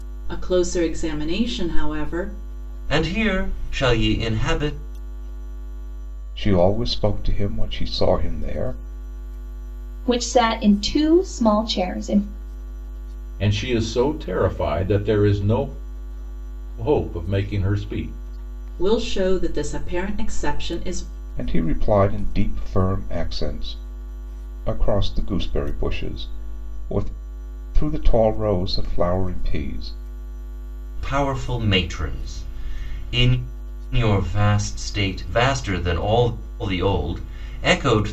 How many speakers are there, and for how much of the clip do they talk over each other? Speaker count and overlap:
5, no overlap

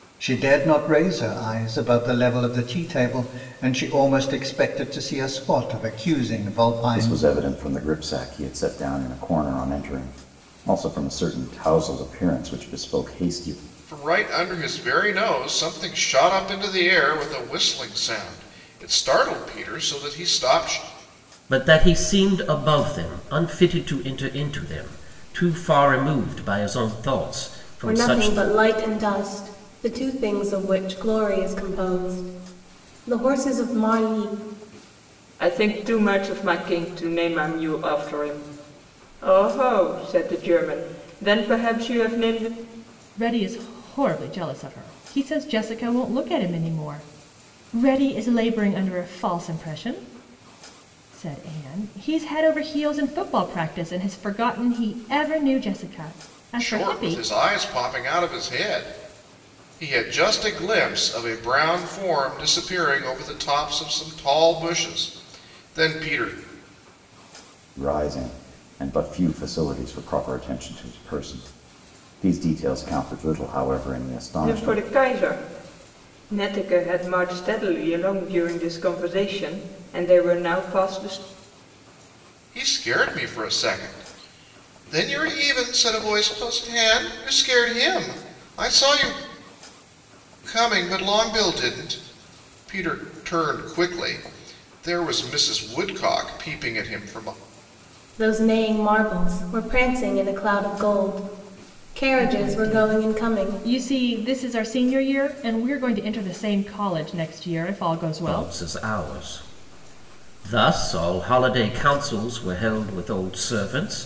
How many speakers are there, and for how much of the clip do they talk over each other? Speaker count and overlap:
7, about 3%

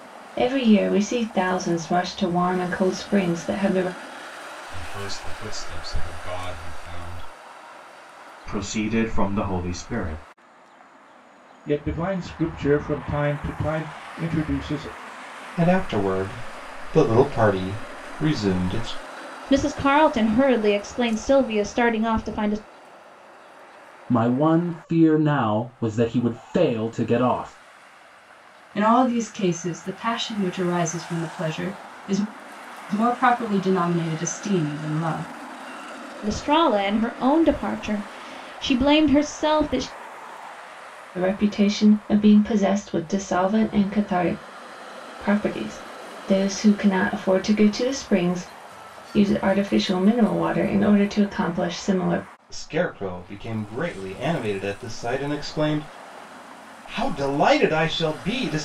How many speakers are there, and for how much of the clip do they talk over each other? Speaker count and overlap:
8, no overlap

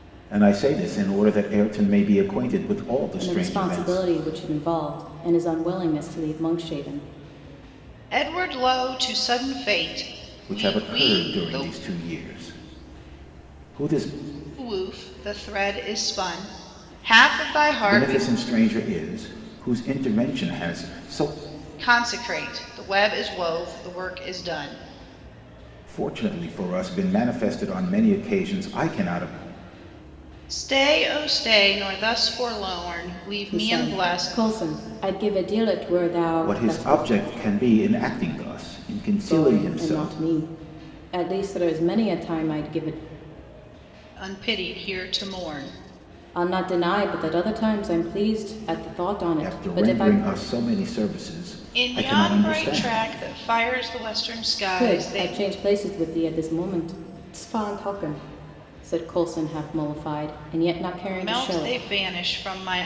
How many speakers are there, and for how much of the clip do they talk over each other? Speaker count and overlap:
3, about 14%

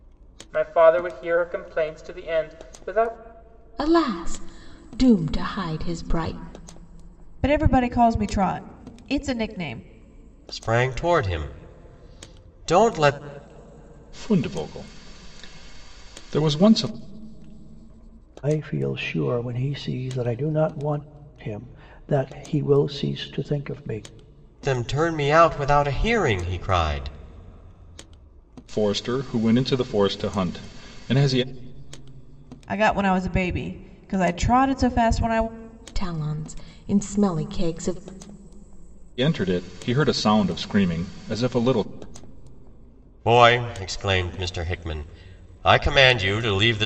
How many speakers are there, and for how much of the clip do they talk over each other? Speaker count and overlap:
6, no overlap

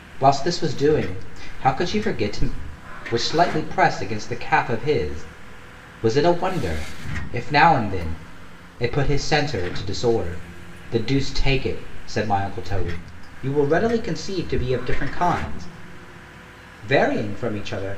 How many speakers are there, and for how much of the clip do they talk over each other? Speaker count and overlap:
1, no overlap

